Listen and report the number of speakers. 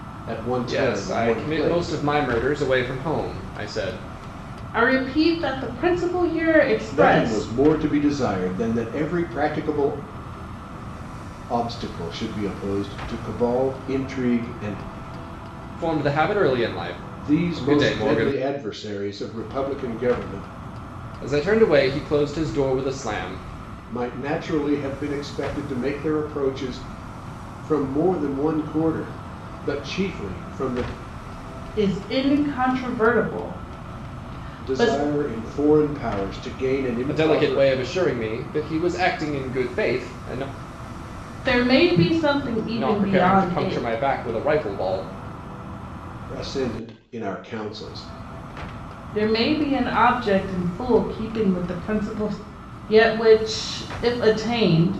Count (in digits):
3